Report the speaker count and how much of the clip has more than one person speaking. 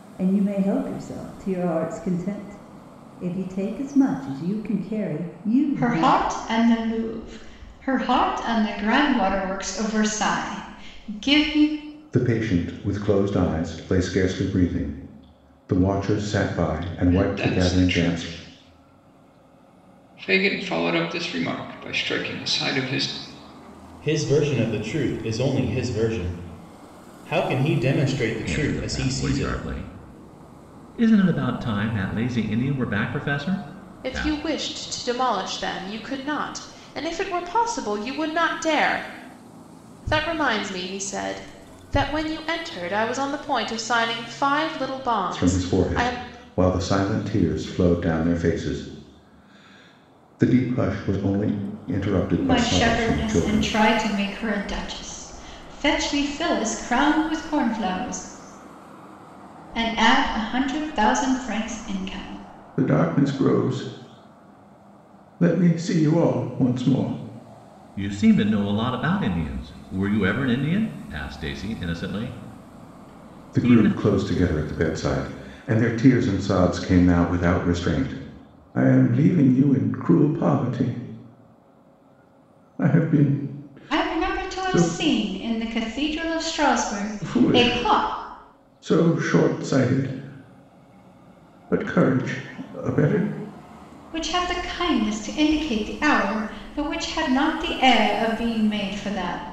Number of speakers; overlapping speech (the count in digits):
7, about 8%